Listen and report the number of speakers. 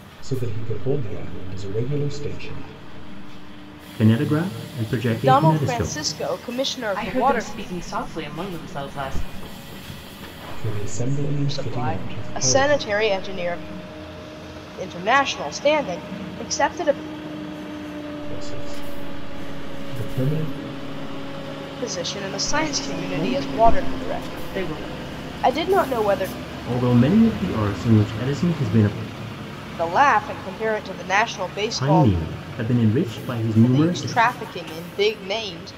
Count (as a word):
four